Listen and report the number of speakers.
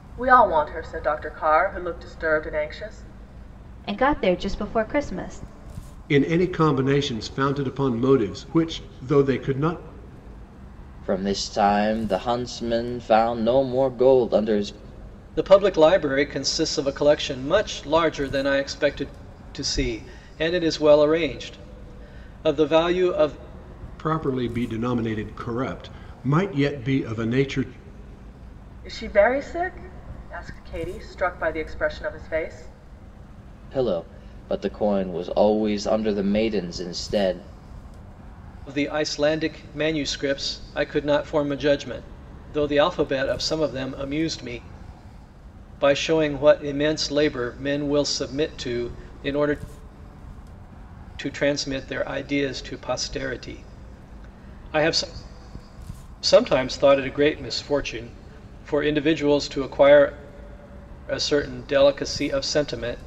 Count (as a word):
five